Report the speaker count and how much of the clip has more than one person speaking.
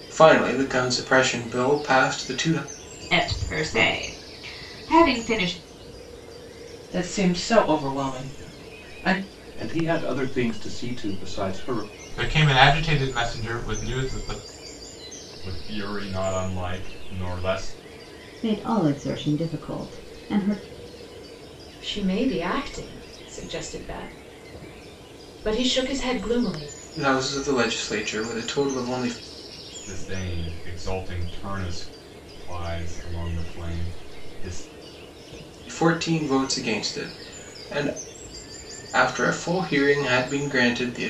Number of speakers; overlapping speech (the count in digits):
8, no overlap